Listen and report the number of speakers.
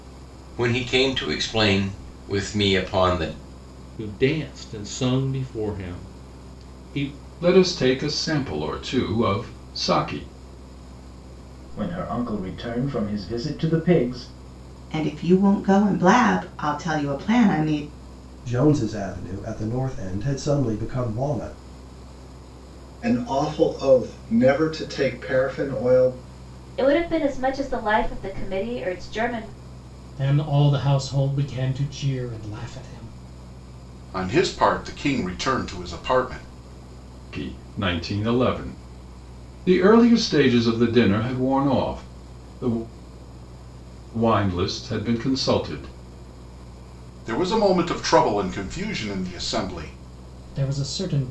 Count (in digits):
10